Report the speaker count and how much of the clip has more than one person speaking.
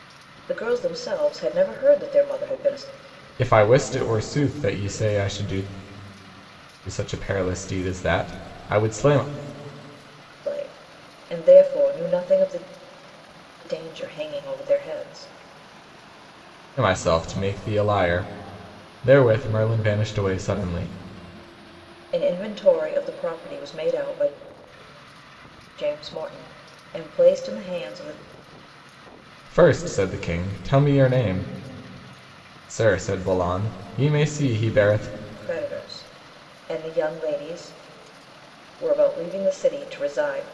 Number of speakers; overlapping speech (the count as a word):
two, no overlap